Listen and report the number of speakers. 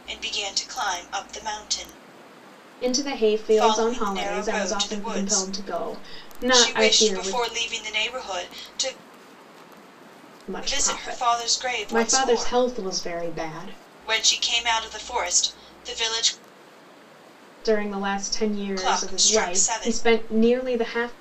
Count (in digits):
2